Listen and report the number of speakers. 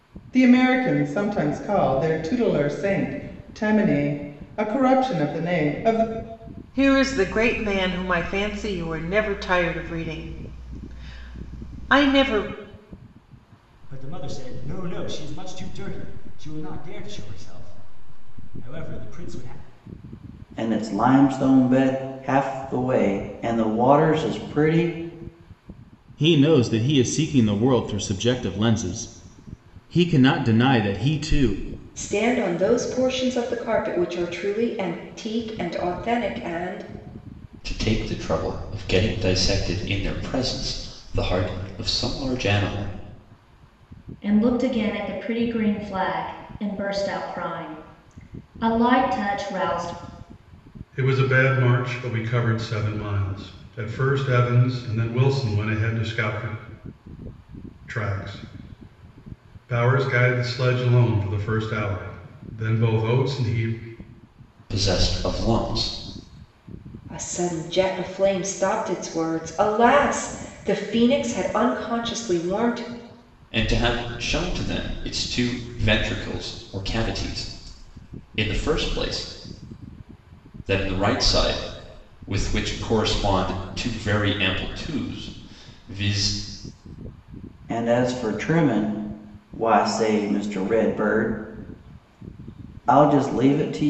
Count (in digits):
9